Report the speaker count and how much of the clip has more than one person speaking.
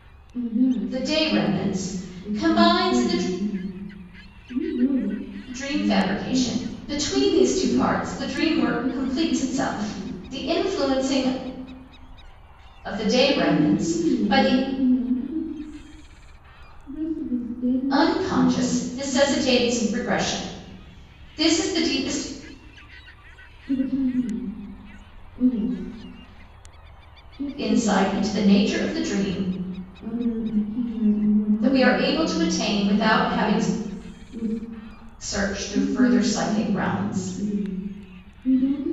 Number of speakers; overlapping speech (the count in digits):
2, about 39%